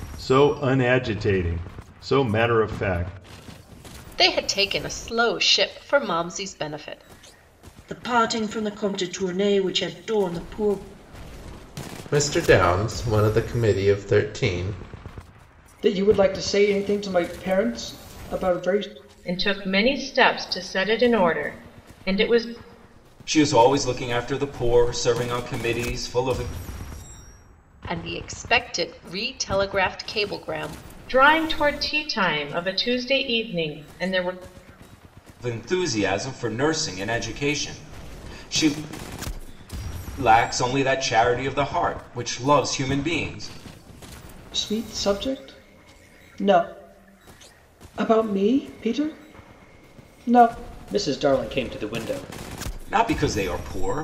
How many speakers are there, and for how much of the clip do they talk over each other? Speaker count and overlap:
7, no overlap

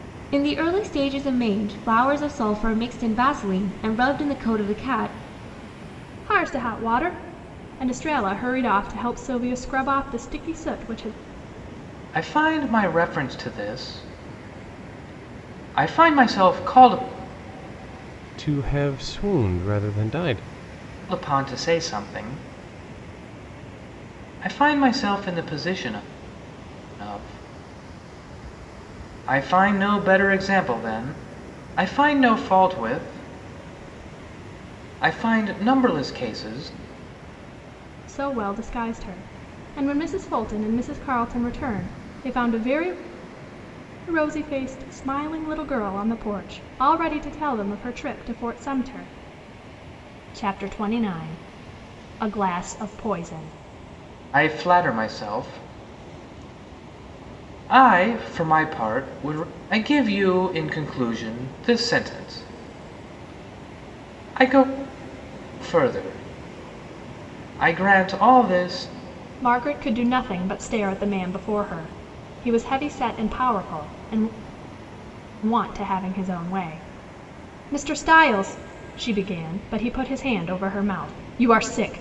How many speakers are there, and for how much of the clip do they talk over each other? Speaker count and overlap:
4, no overlap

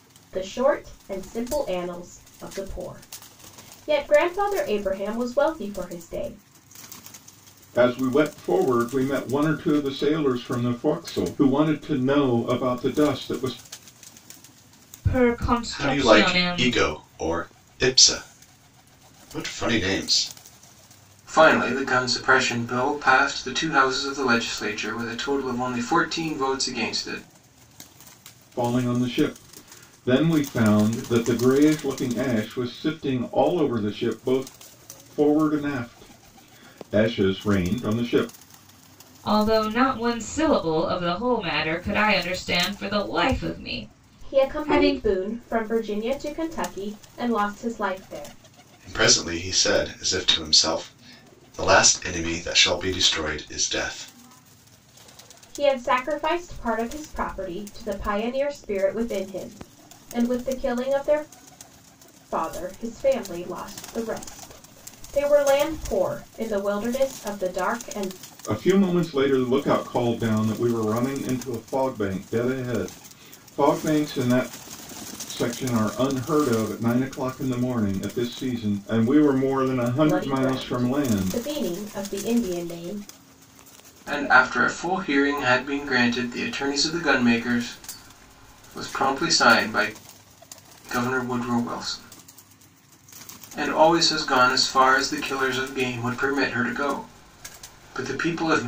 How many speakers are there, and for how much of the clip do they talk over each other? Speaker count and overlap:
5, about 3%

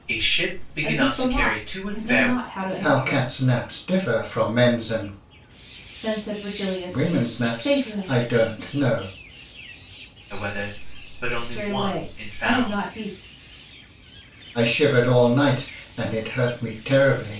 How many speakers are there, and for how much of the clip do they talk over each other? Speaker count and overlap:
3, about 27%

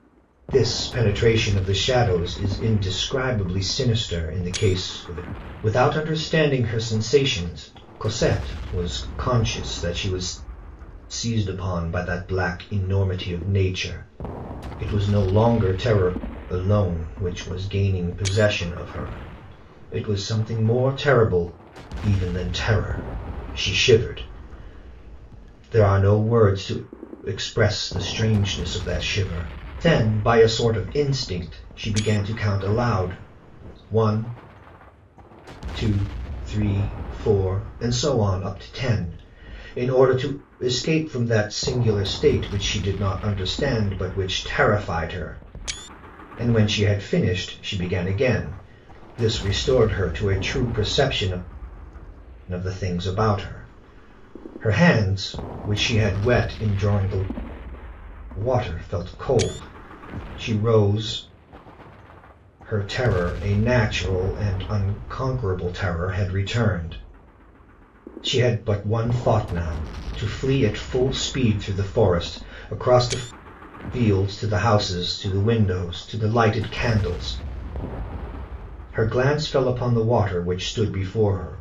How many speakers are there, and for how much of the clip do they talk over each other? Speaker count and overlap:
1, no overlap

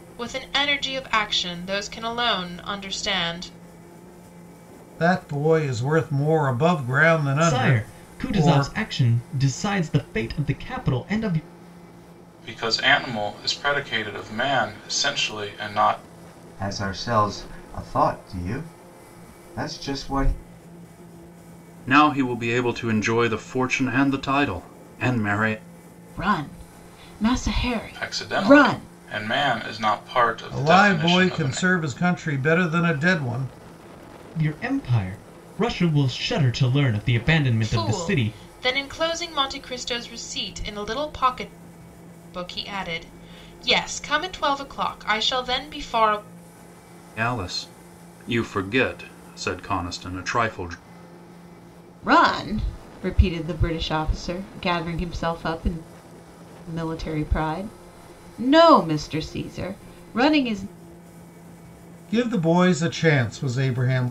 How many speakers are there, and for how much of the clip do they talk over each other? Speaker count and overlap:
7, about 6%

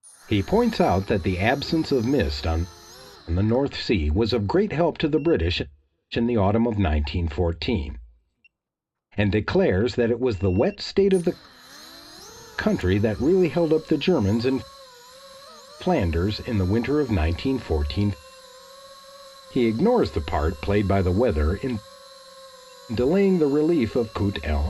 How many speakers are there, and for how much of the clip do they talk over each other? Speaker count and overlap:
1, no overlap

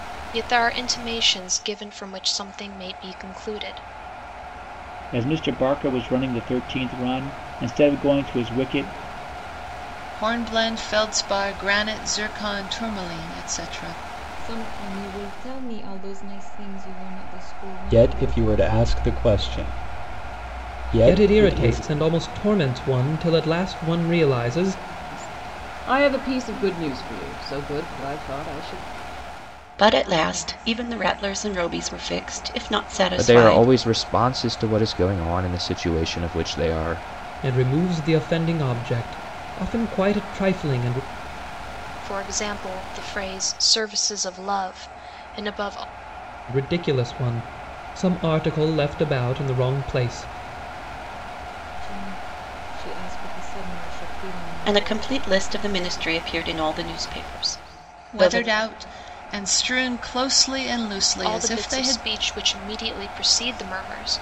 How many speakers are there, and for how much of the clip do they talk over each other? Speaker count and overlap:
9, about 6%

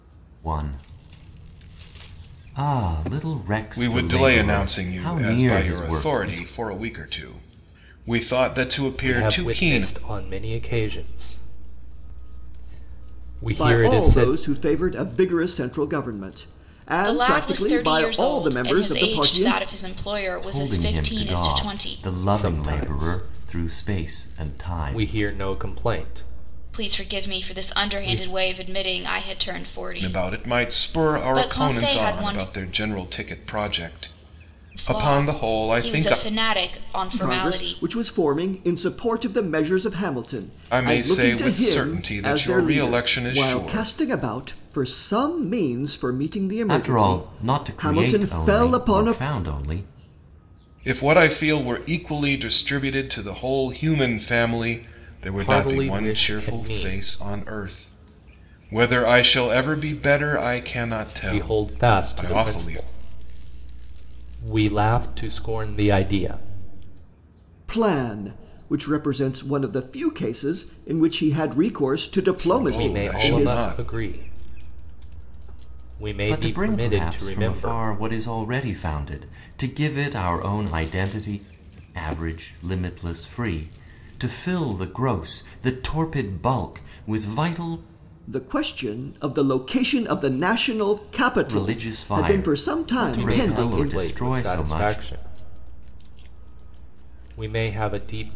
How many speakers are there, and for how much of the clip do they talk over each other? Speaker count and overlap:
5, about 34%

